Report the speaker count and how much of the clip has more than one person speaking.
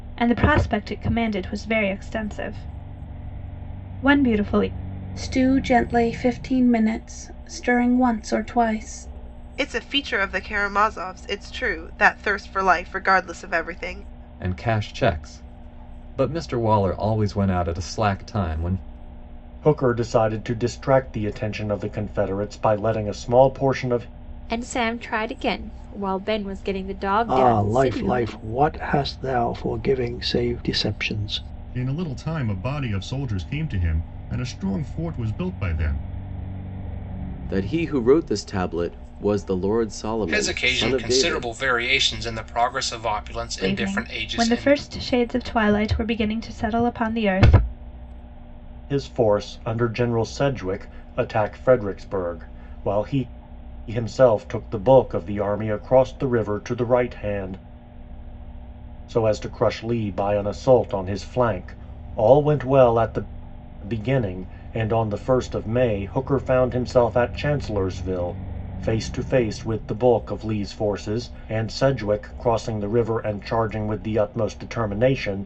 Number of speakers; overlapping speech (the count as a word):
ten, about 5%